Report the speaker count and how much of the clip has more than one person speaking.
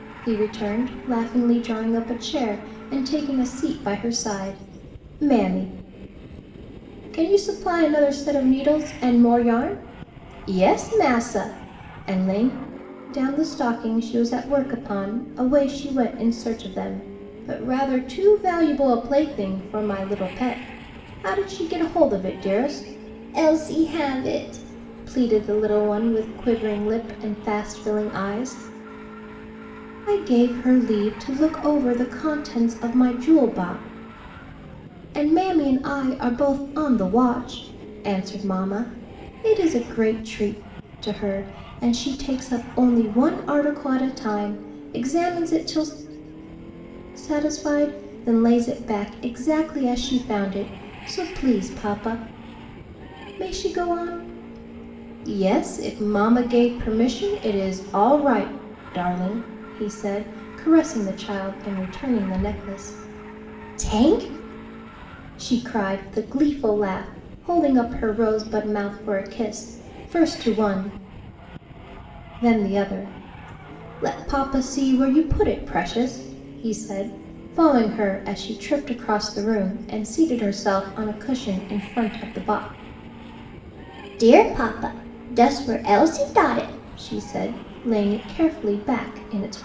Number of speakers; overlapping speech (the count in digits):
1, no overlap